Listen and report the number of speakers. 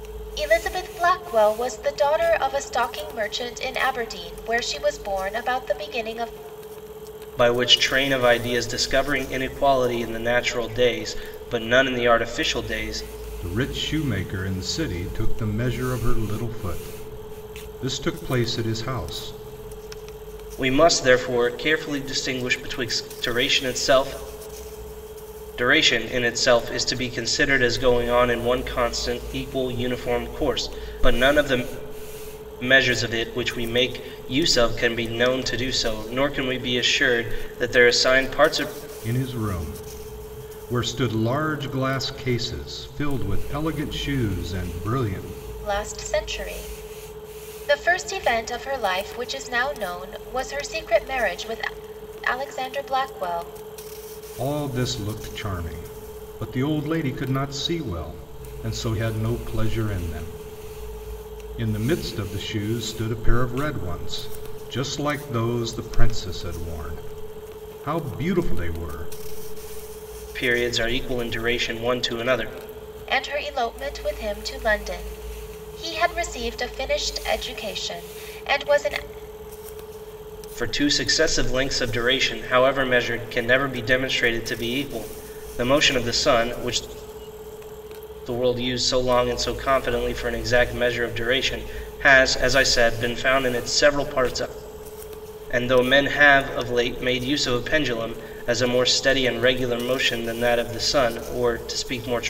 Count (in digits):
3